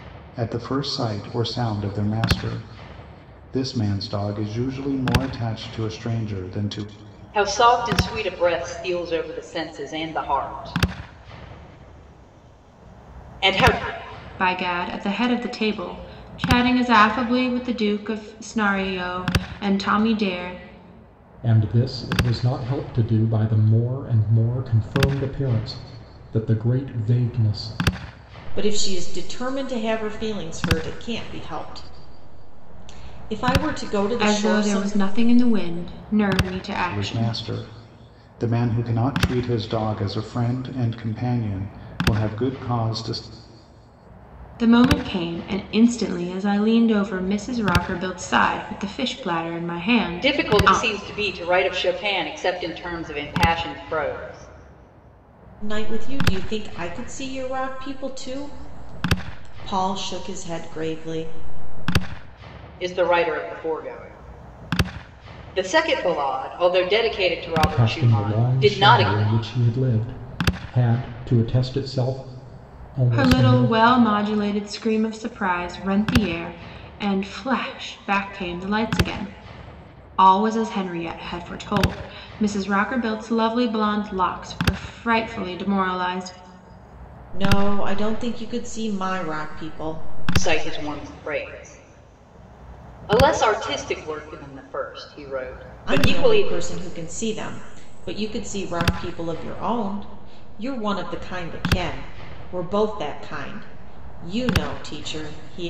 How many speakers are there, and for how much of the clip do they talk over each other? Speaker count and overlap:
5, about 5%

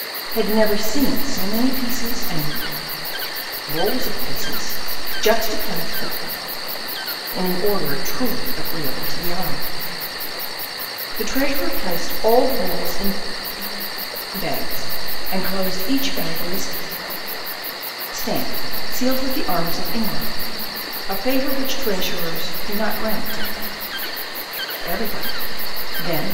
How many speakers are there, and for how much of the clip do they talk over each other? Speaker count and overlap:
1, no overlap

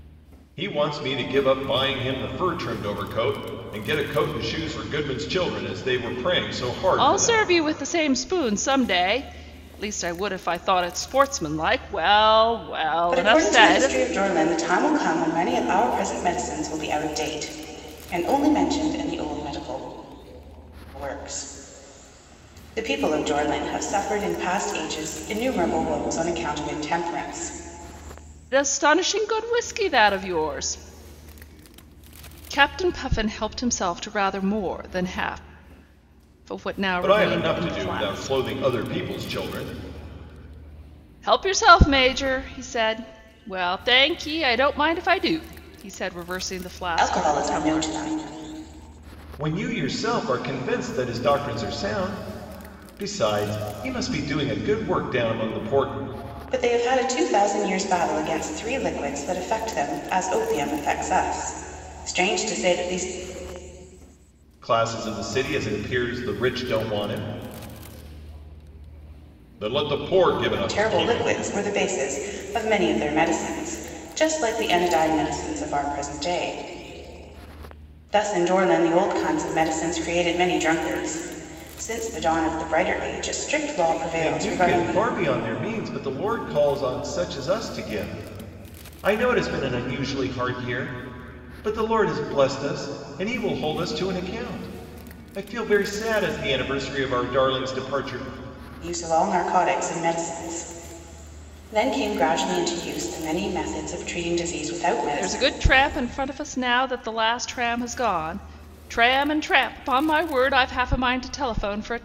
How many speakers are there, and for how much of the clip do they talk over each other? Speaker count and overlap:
3, about 5%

